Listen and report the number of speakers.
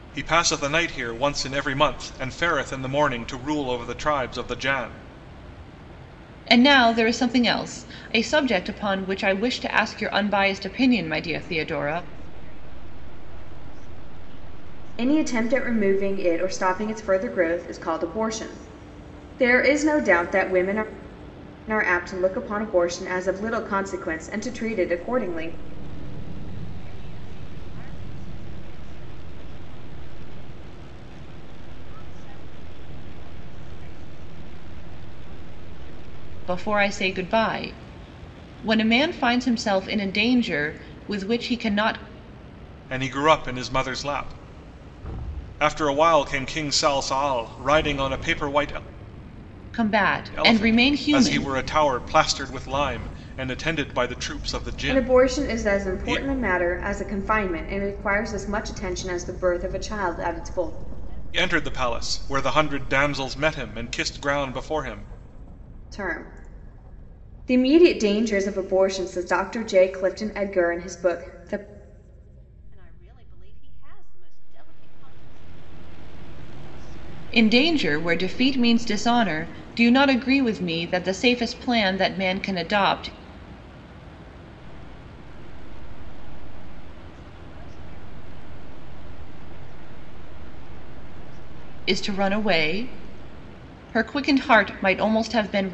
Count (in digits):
4